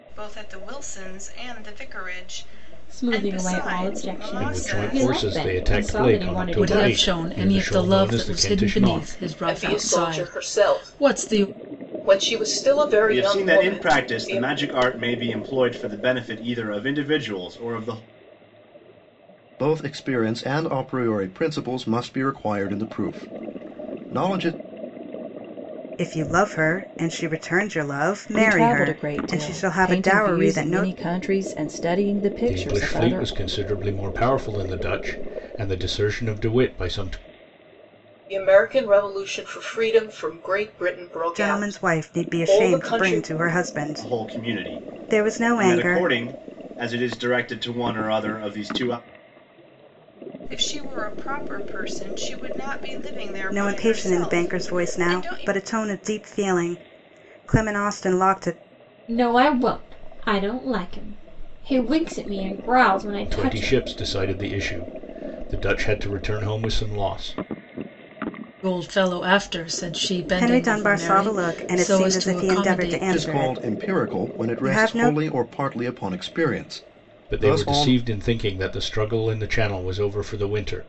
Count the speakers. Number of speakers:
9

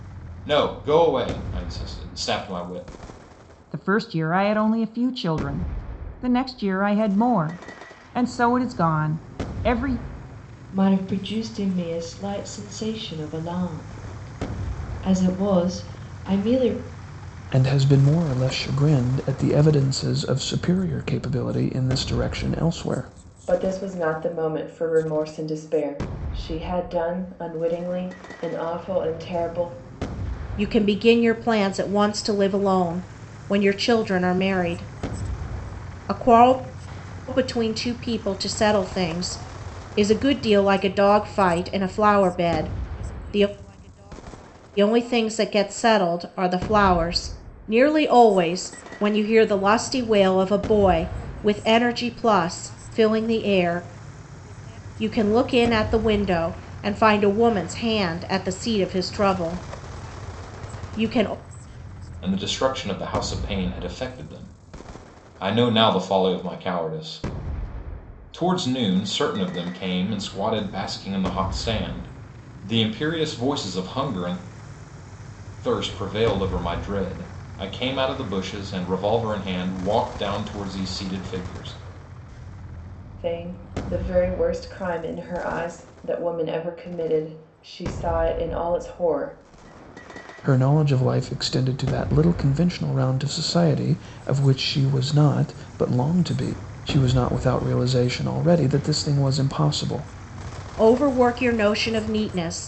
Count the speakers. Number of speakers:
6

